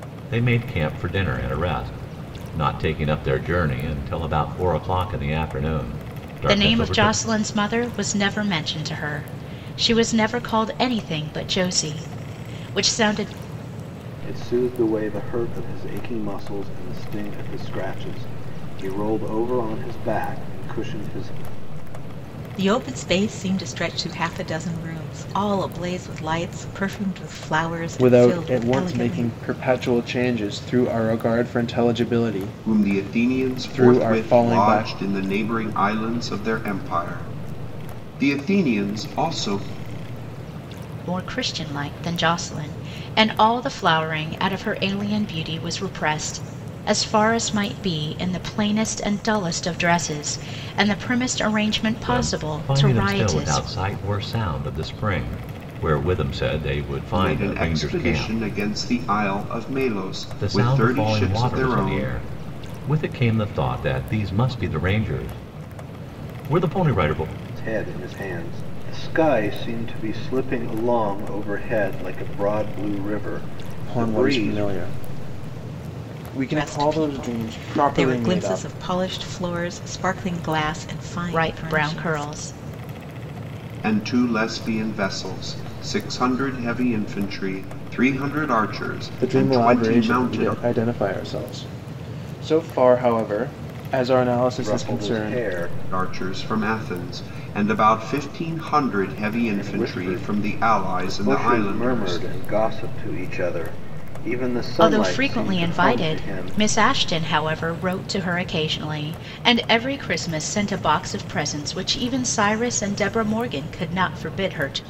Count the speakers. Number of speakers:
six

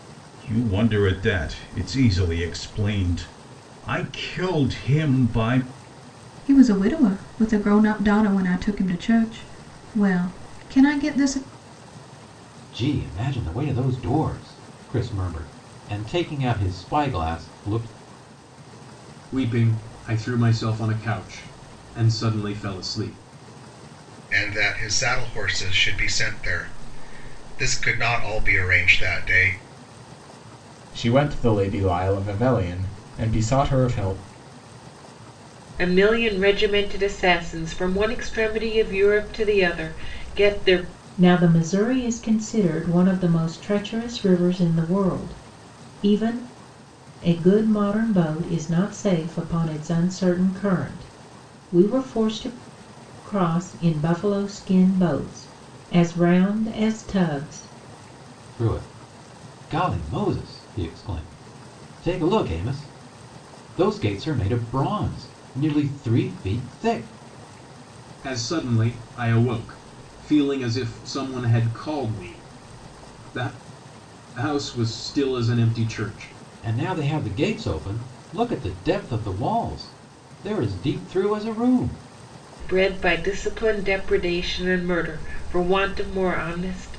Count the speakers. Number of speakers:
eight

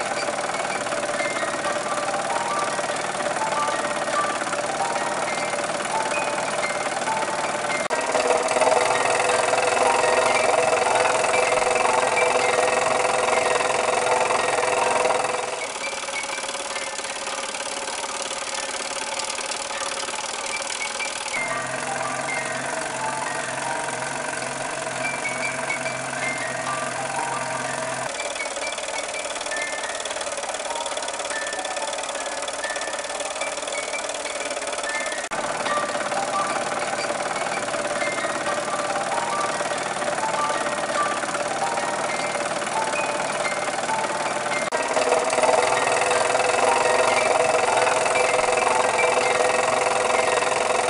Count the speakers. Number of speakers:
zero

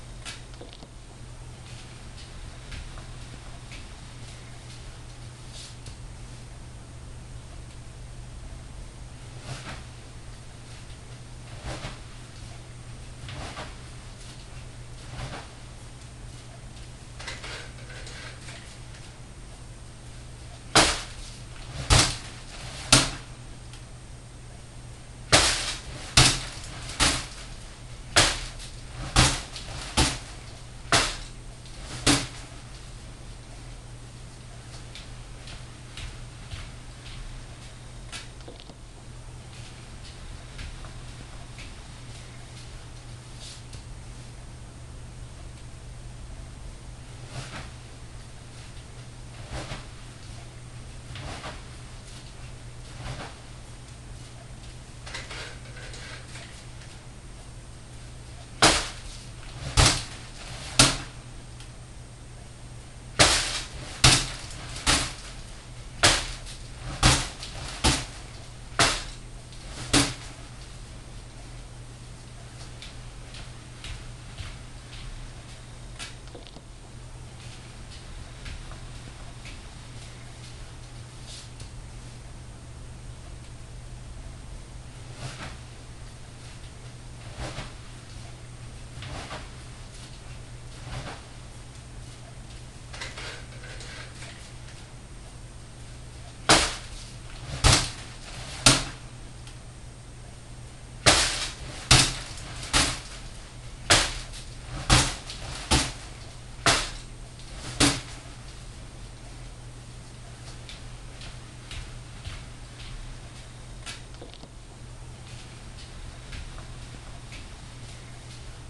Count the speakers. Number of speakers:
zero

